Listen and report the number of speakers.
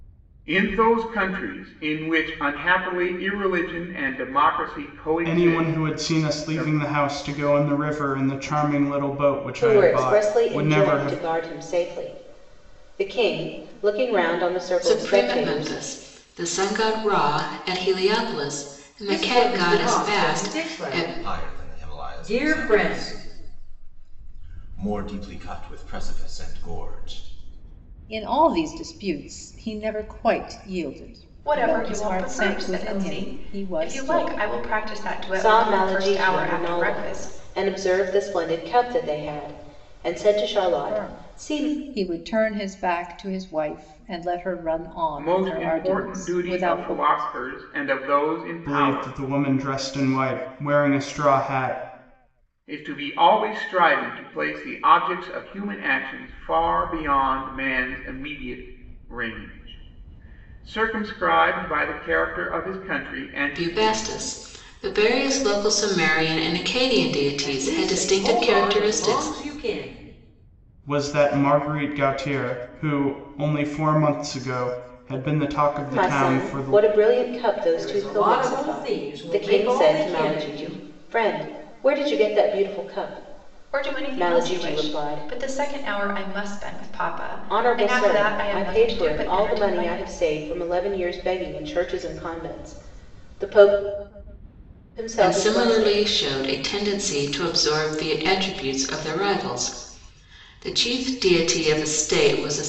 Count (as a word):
eight